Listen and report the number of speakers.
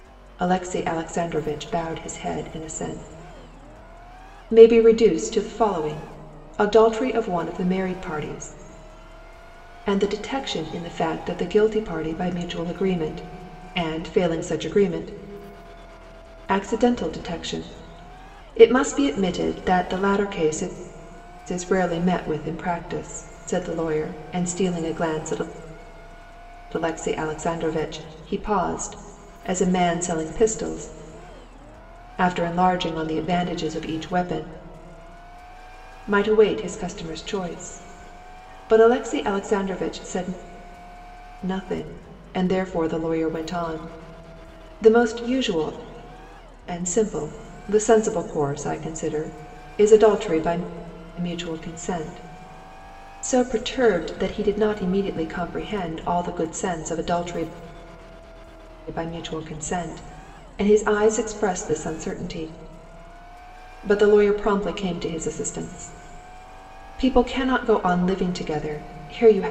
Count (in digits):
1